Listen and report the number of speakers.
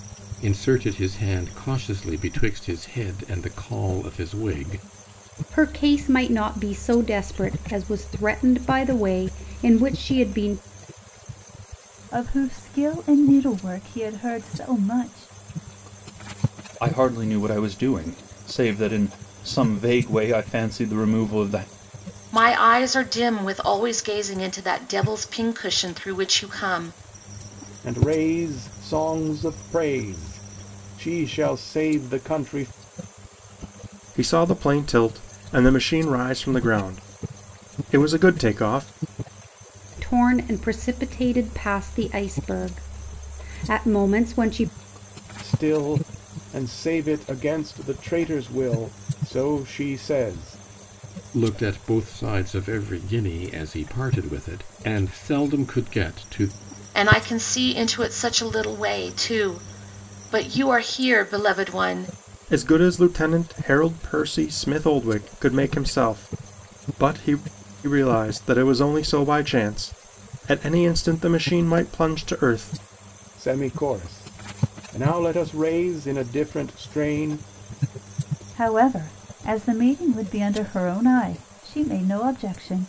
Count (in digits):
7